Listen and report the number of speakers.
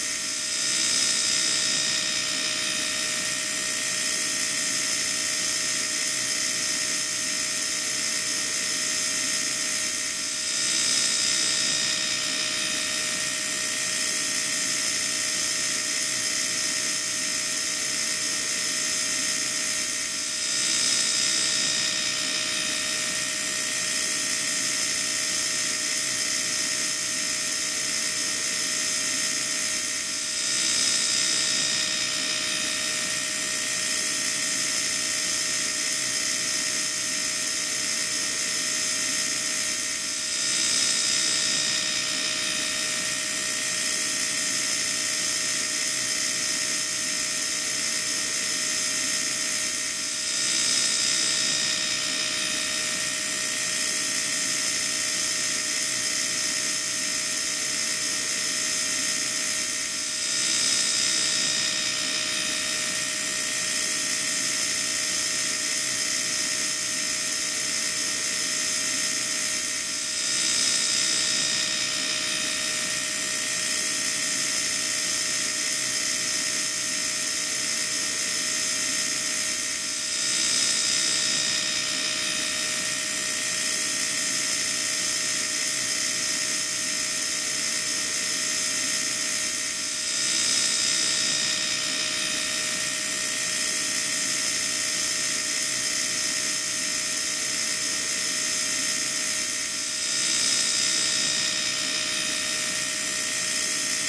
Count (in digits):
0